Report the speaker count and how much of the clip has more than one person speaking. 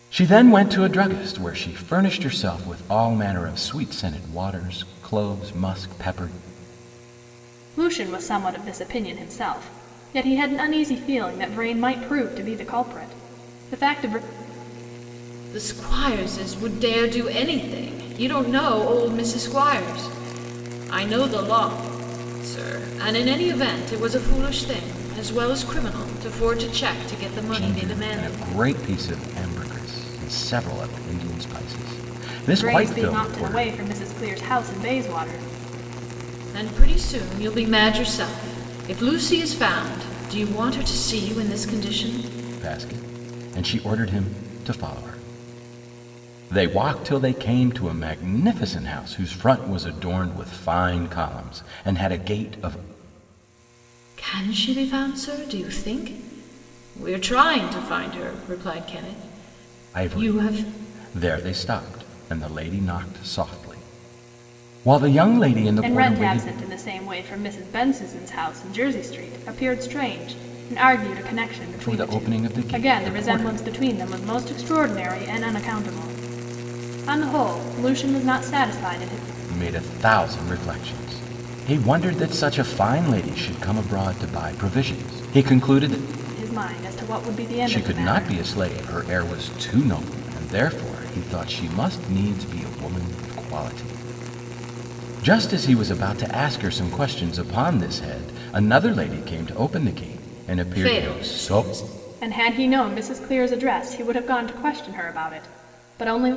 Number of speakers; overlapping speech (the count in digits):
3, about 6%